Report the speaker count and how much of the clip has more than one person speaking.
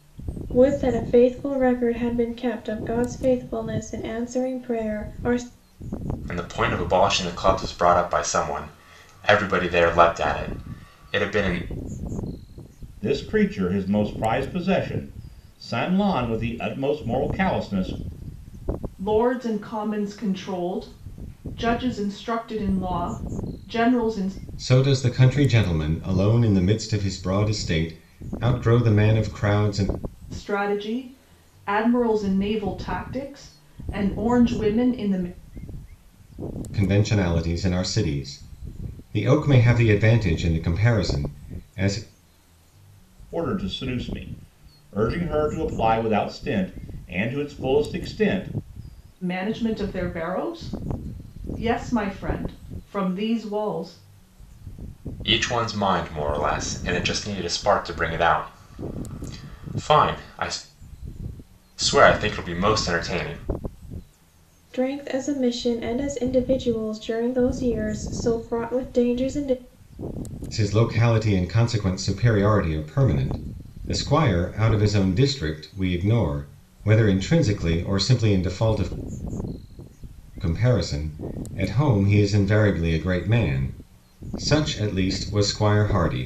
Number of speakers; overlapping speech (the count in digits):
5, no overlap